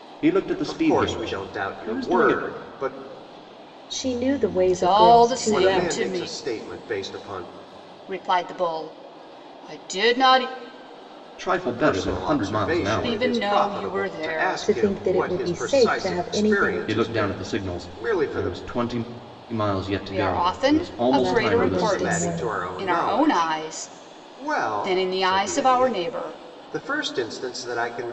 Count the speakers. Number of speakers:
four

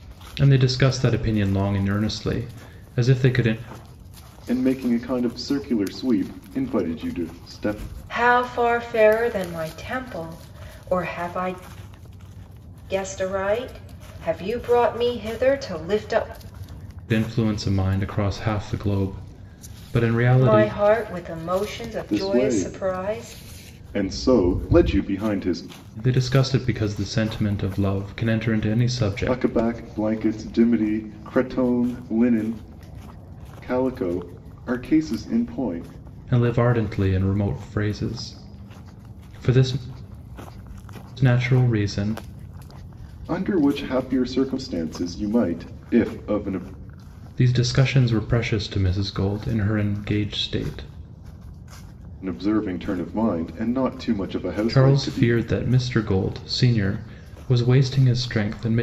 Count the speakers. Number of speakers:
three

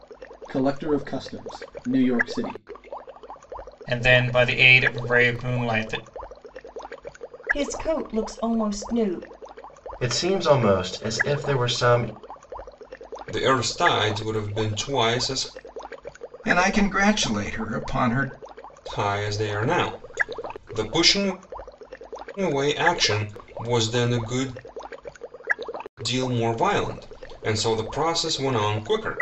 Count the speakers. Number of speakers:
six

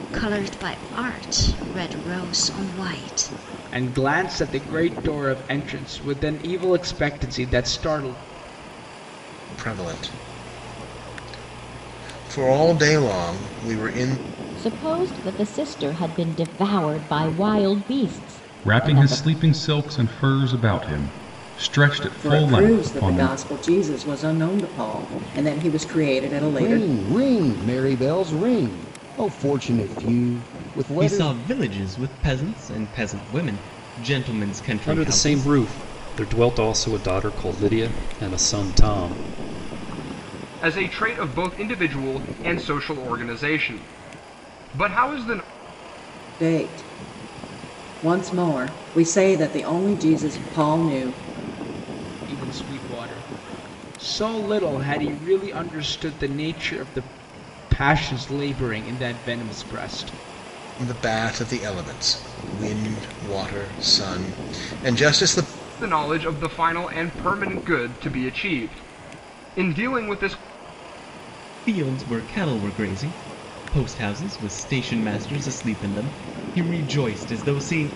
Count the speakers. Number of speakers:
ten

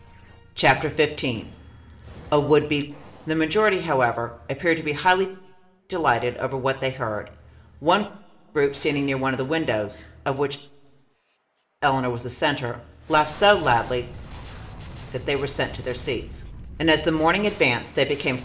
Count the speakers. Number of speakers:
one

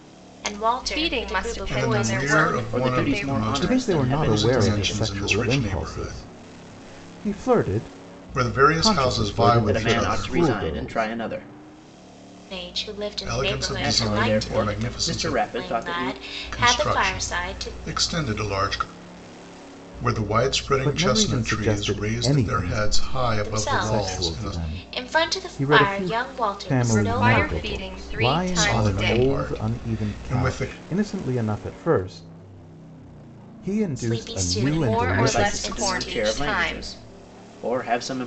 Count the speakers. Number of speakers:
five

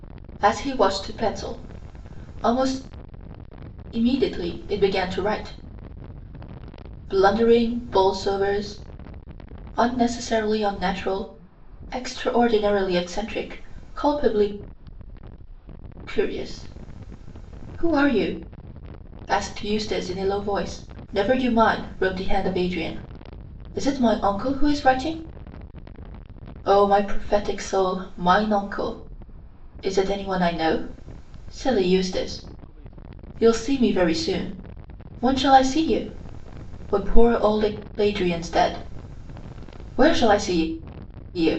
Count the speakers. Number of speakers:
one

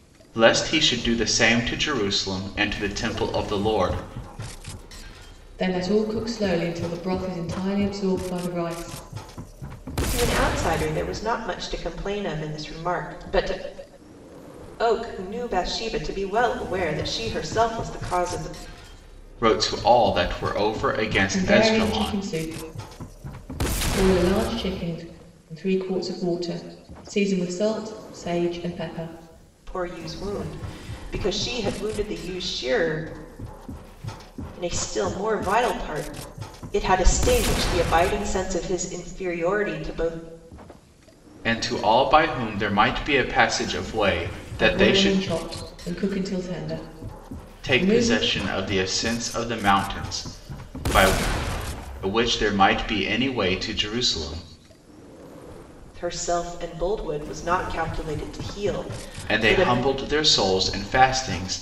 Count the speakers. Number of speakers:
three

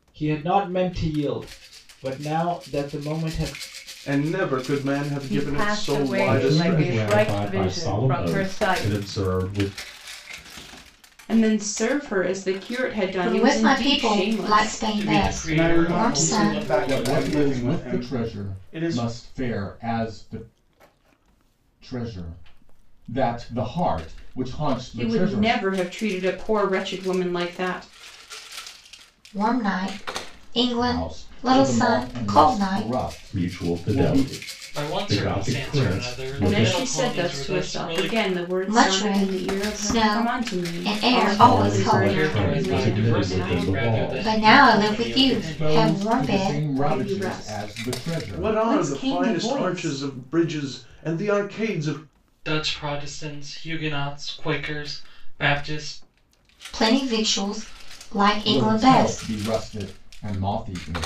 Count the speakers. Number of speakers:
nine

